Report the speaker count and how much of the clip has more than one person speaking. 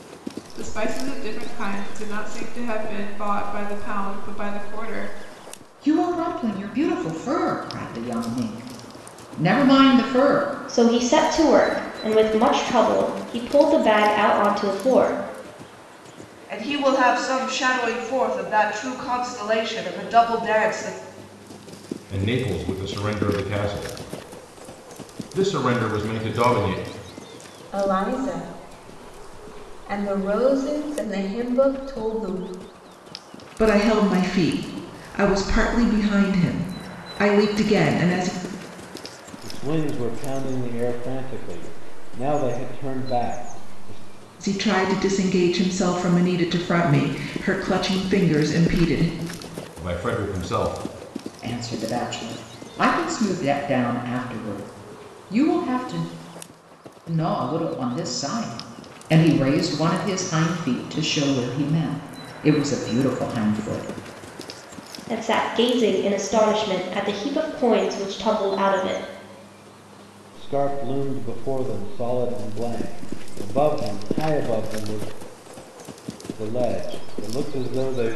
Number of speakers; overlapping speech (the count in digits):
8, no overlap